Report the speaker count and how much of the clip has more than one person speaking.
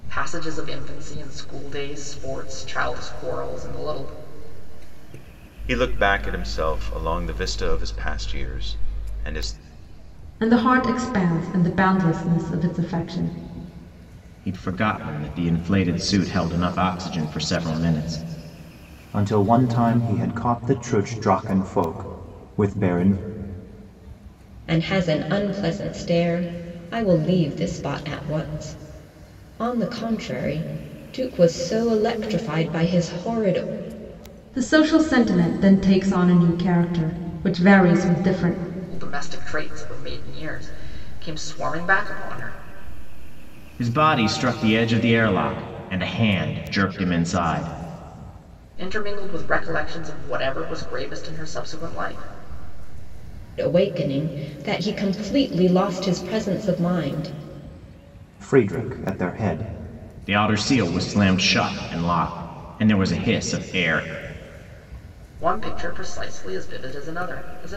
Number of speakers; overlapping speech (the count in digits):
6, no overlap